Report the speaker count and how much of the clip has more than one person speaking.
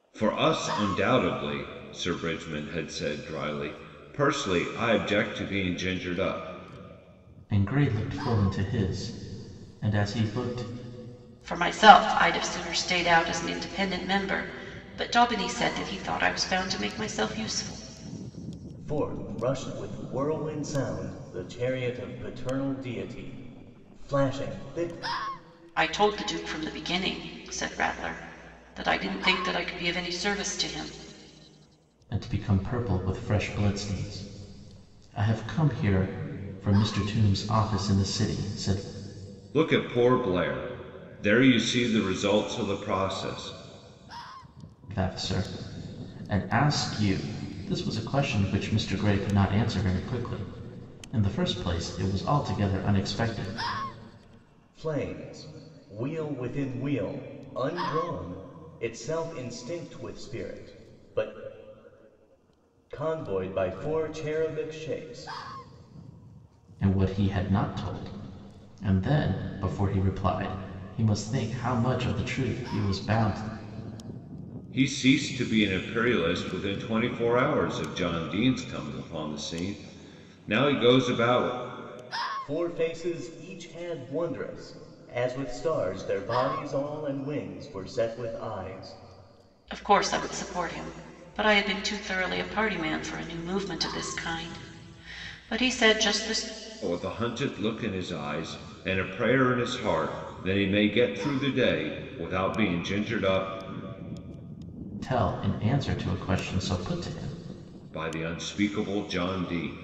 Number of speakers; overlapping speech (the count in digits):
4, no overlap